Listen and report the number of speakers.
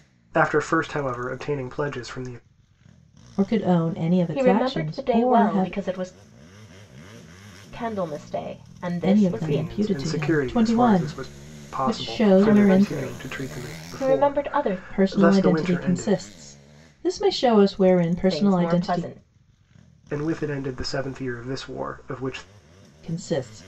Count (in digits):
3